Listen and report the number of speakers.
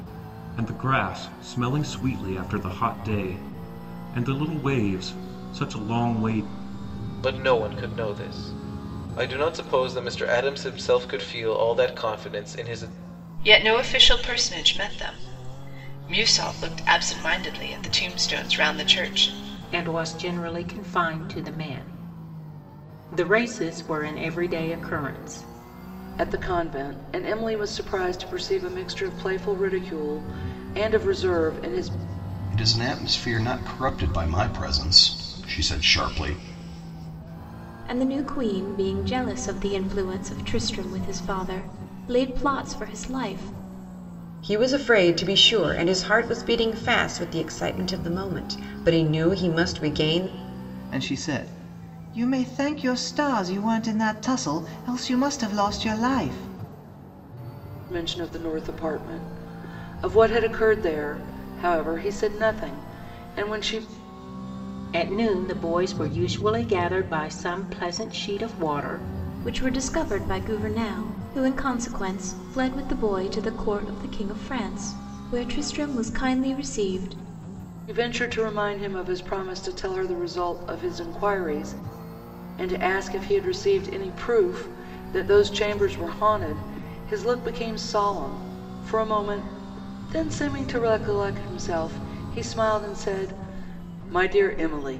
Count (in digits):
9